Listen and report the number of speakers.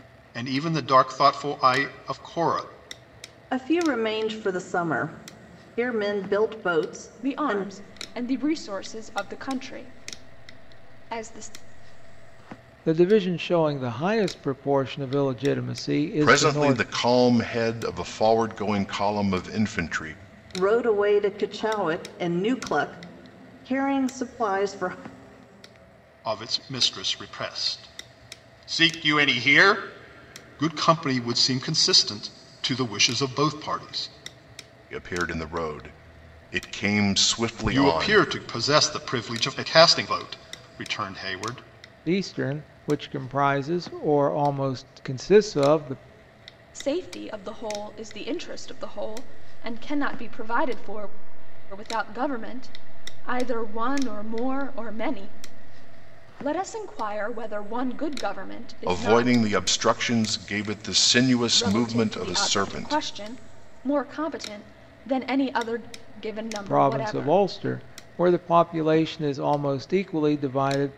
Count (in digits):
5